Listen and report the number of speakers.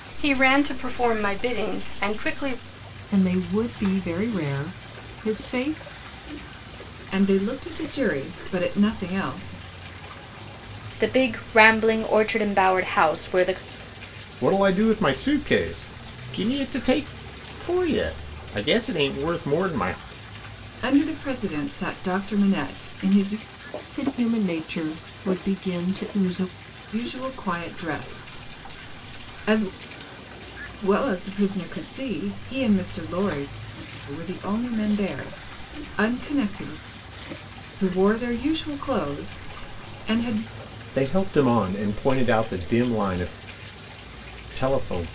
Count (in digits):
5